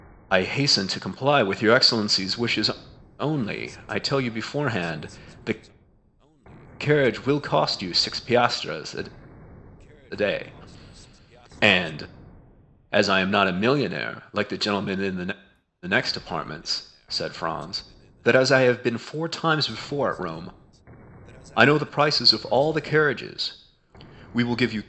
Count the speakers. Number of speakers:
1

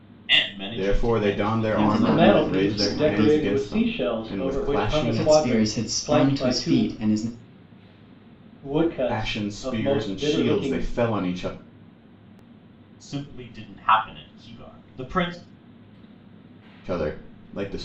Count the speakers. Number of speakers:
4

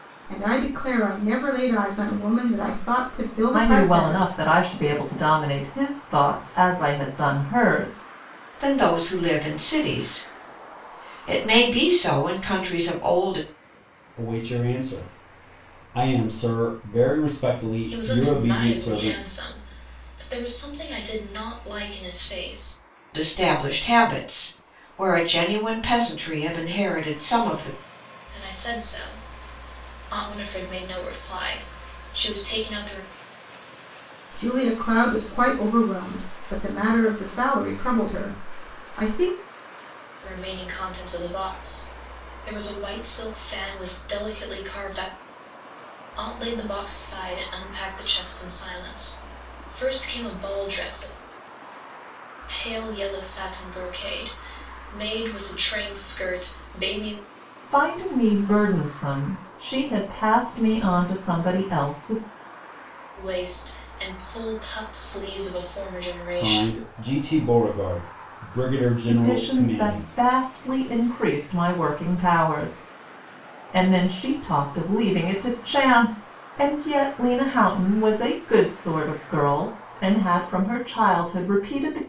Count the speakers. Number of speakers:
5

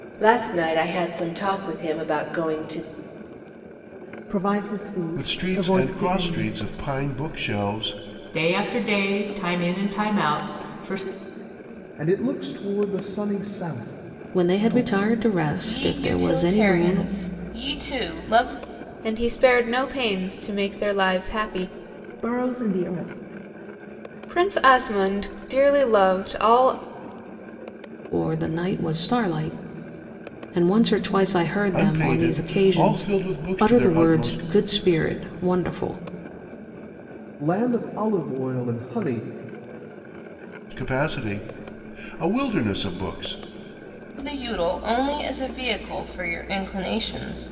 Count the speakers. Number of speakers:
8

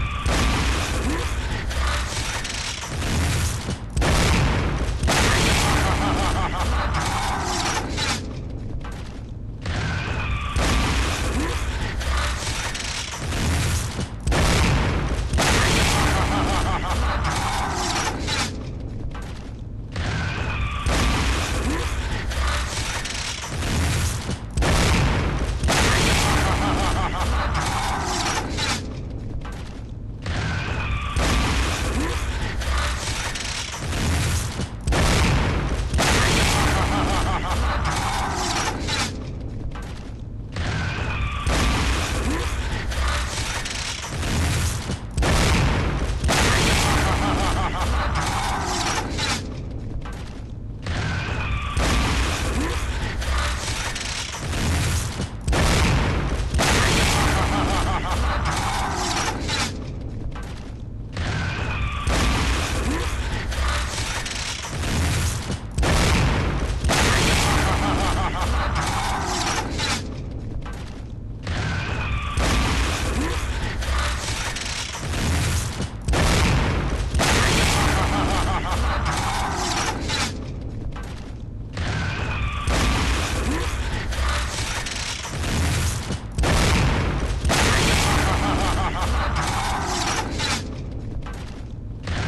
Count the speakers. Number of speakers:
0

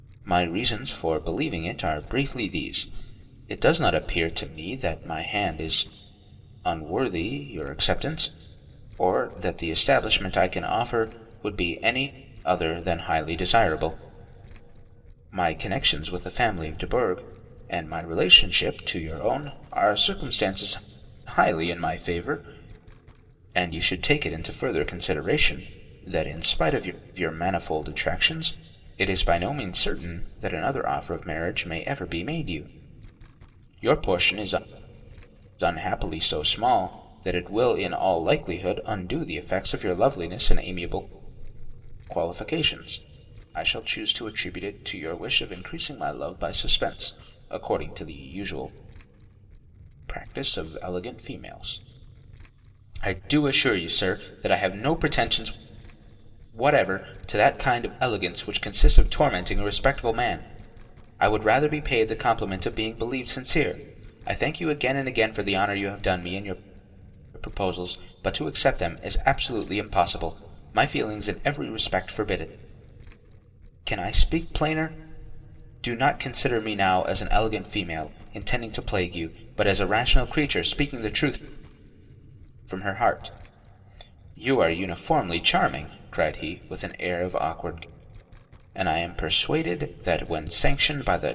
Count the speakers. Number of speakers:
1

